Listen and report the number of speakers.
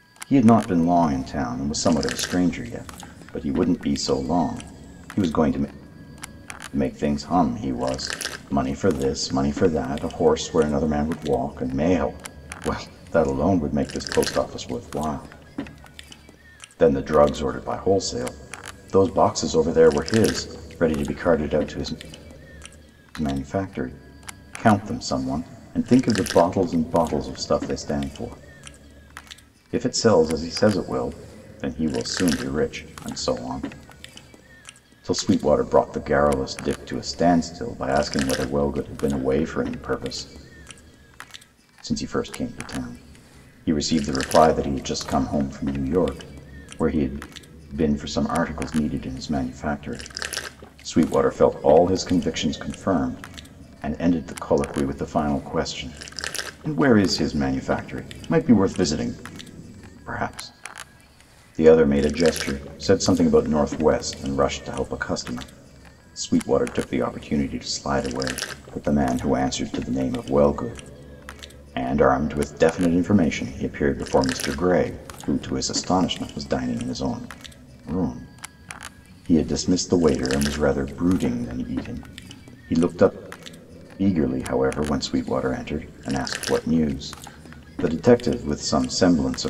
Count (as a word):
one